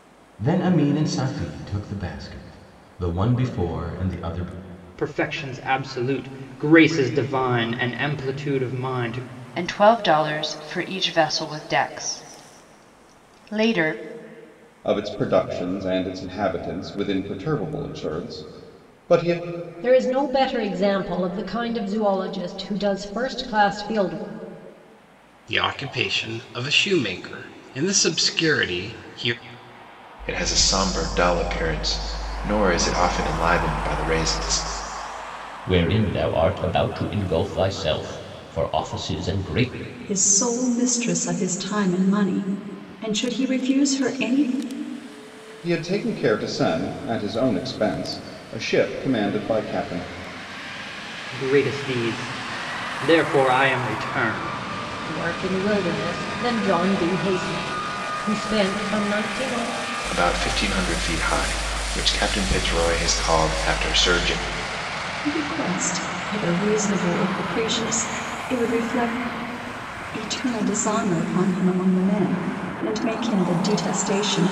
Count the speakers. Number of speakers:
9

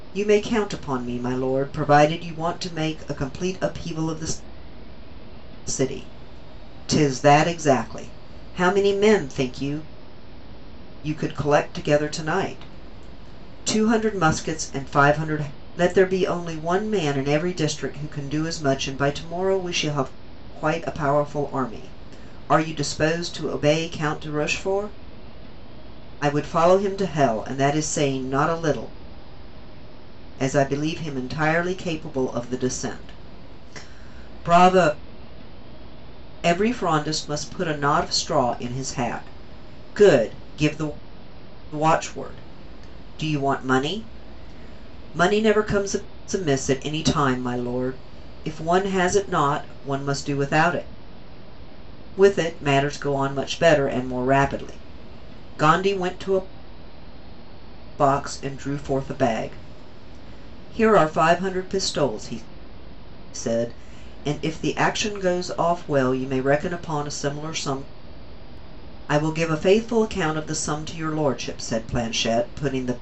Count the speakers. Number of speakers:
1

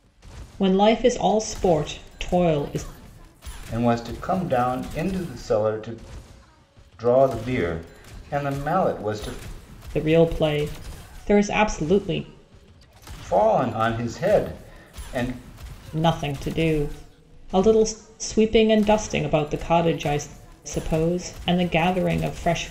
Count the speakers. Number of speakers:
2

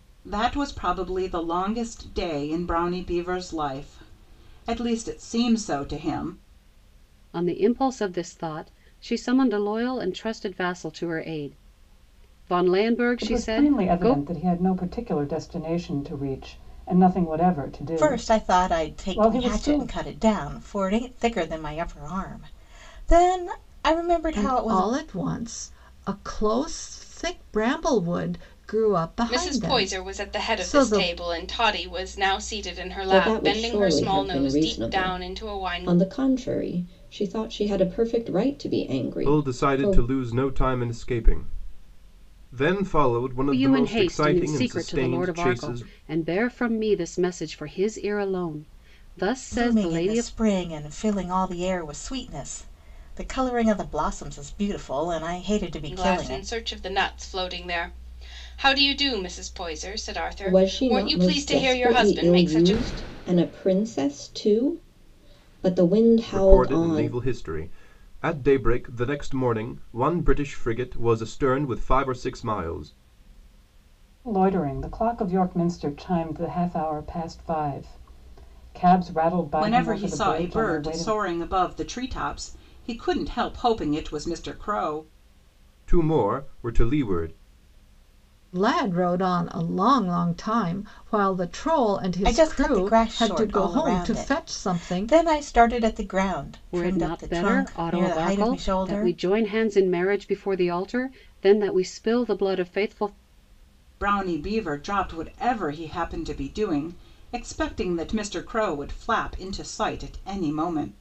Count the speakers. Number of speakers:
8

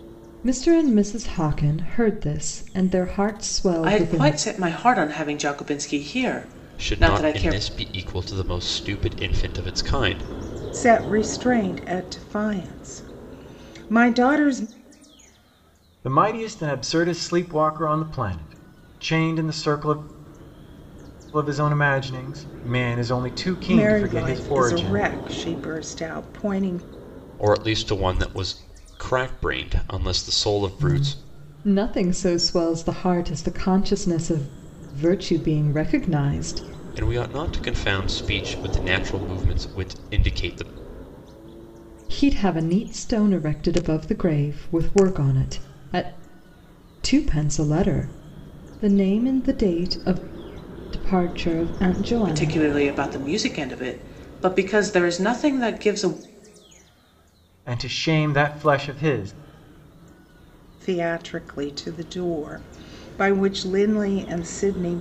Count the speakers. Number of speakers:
5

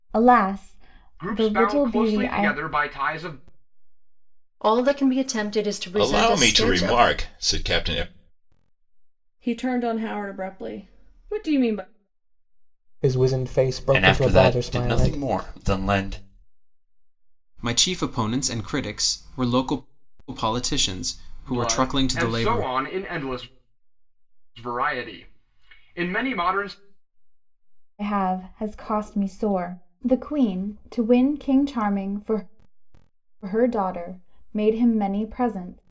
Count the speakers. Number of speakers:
8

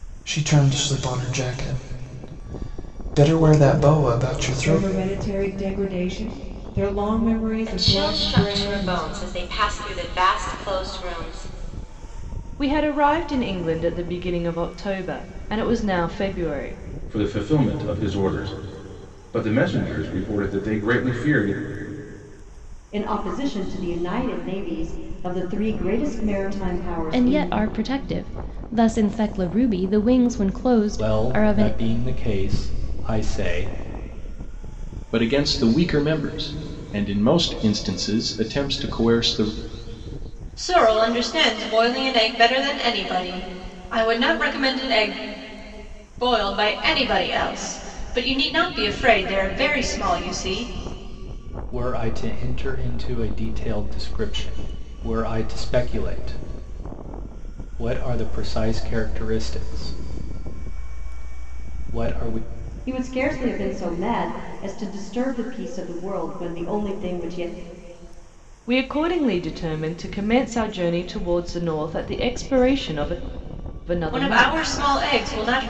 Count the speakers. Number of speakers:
10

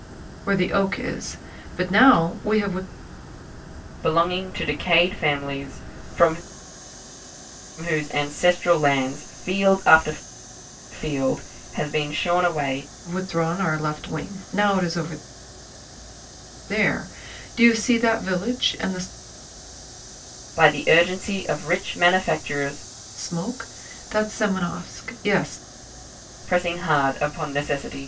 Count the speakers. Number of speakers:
2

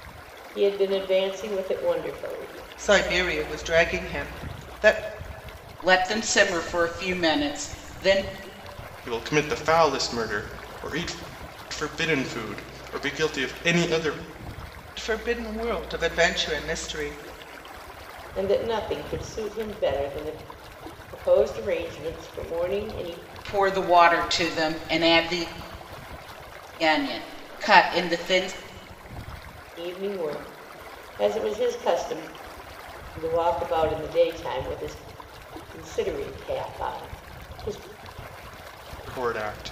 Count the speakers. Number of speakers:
4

